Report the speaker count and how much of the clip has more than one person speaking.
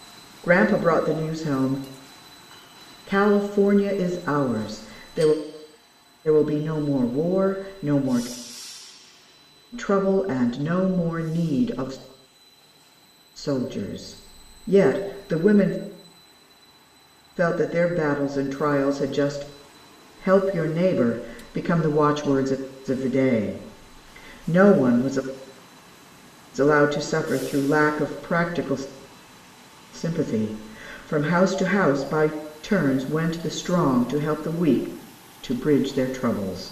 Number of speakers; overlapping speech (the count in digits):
1, no overlap